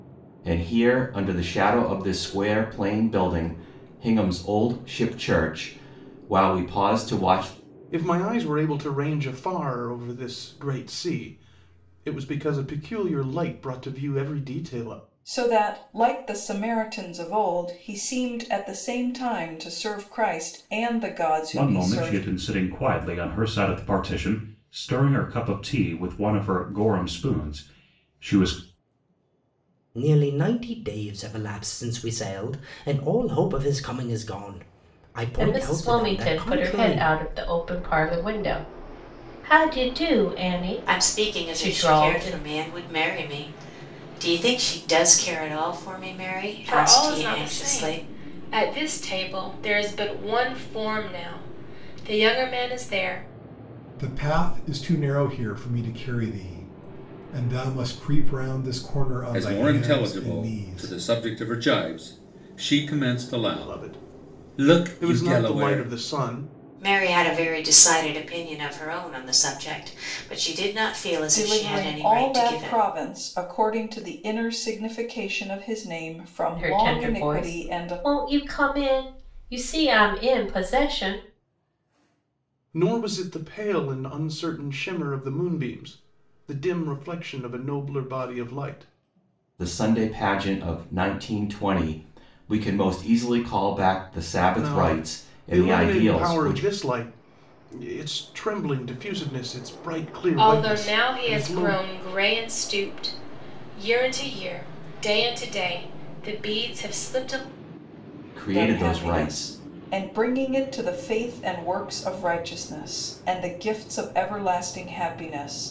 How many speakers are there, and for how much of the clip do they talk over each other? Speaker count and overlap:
10, about 15%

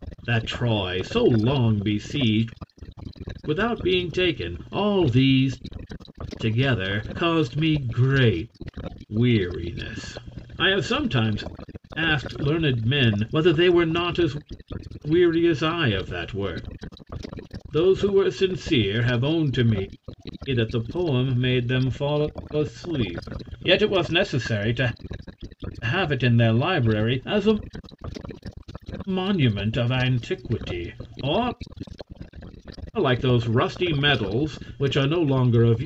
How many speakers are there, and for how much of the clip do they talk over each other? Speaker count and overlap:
1, no overlap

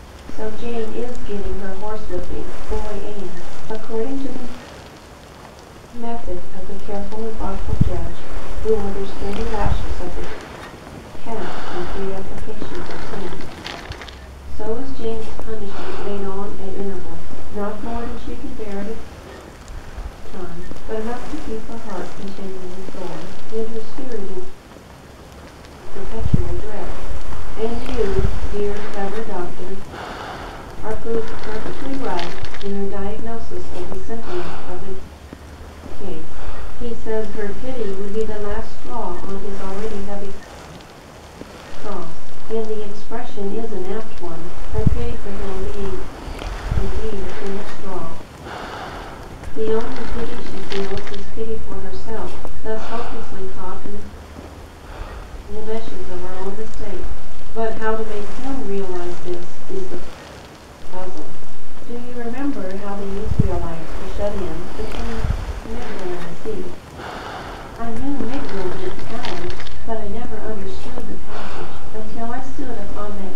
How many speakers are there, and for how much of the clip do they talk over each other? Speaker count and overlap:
1, no overlap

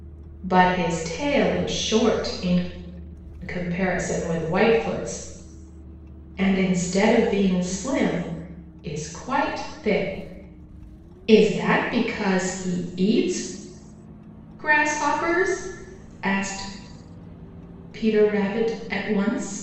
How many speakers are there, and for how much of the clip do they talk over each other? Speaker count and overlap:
1, no overlap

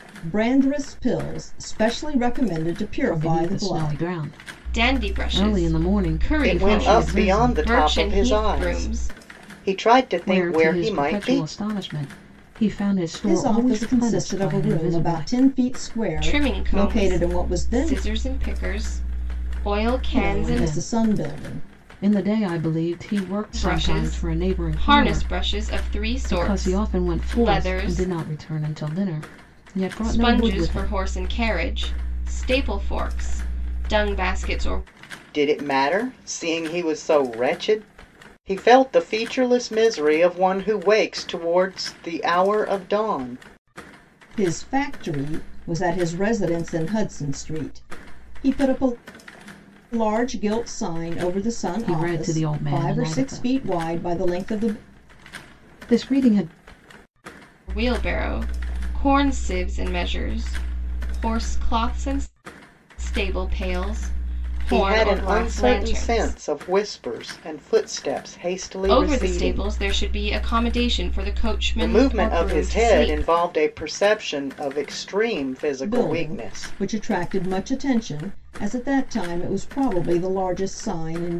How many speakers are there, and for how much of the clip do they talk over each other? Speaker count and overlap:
4, about 31%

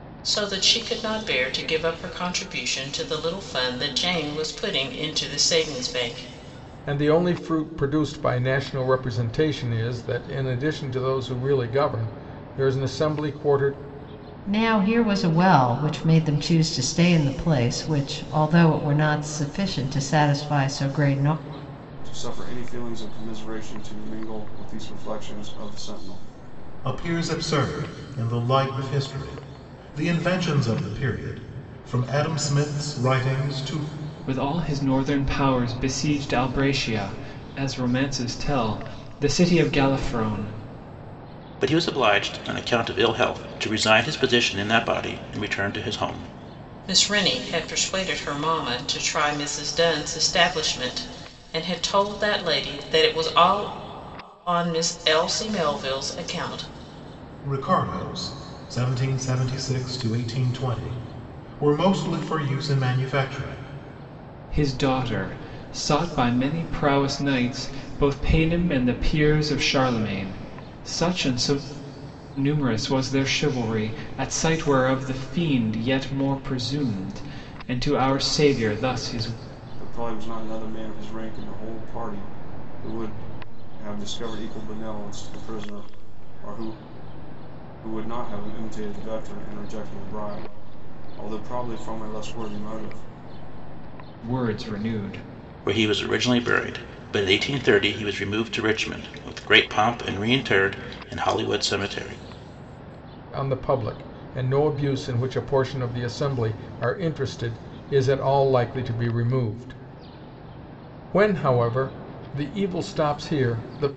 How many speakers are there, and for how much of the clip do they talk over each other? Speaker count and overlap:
7, no overlap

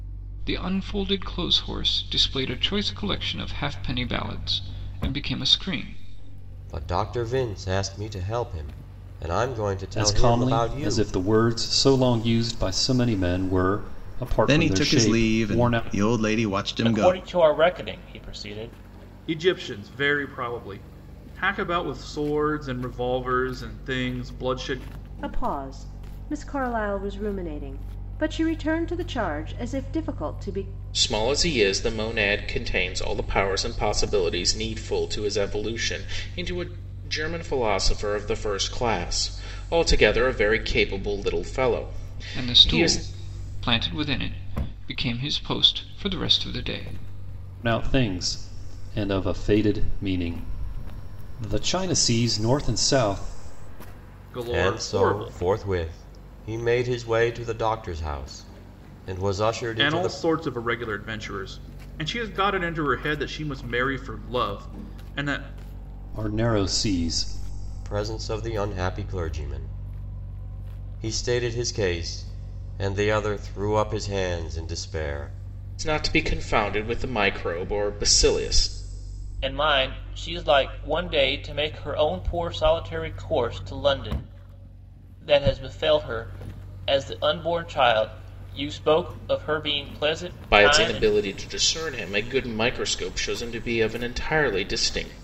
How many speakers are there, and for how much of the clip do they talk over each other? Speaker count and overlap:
8, about 6%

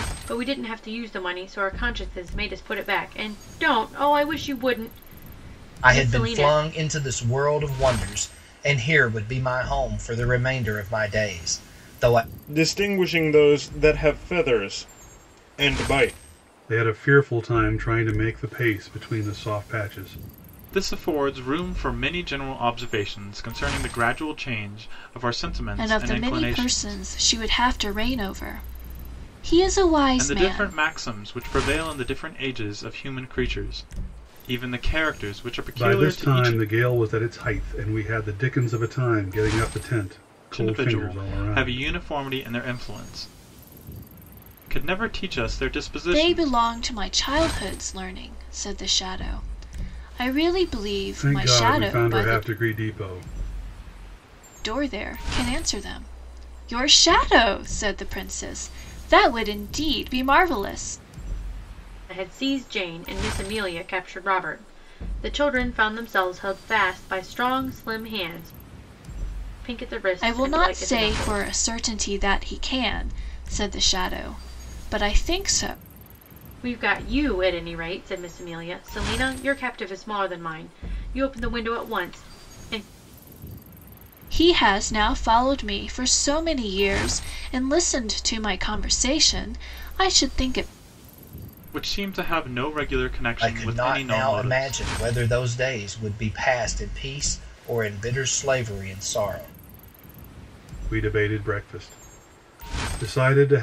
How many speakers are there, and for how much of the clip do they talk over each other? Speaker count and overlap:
6, about 9%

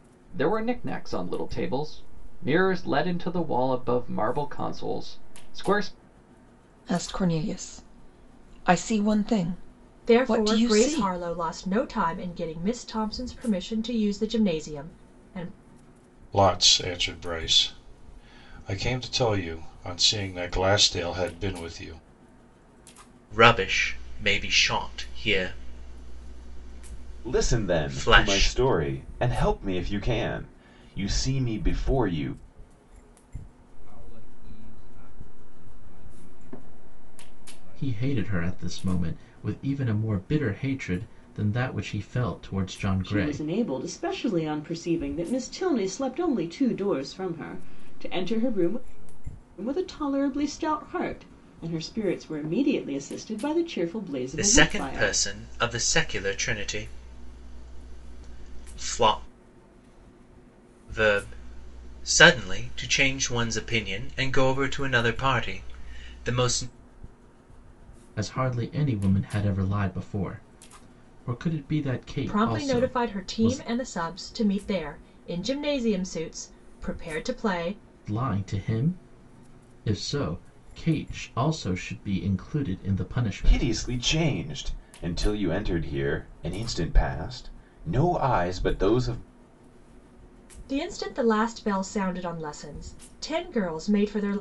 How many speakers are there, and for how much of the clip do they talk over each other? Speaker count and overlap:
9, about 9%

